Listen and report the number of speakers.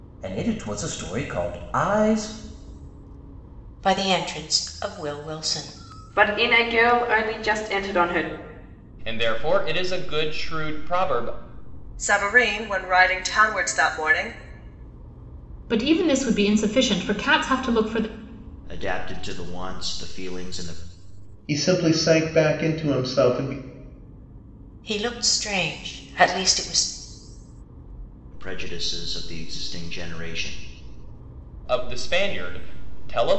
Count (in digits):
8